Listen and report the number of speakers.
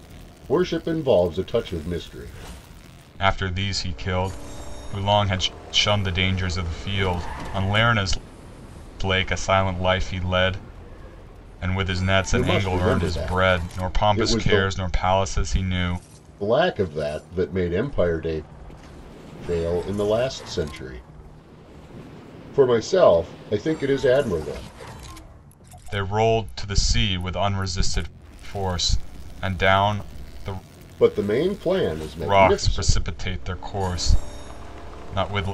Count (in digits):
2